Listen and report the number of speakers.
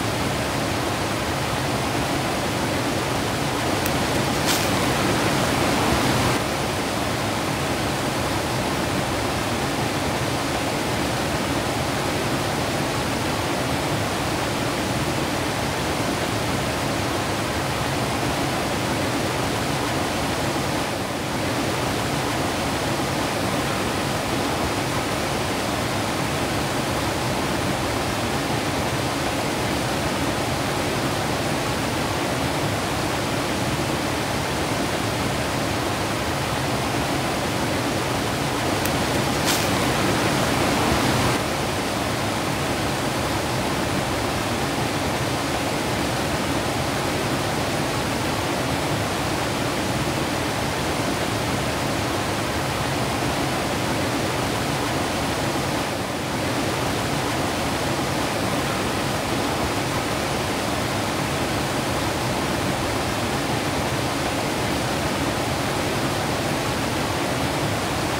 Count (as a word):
zero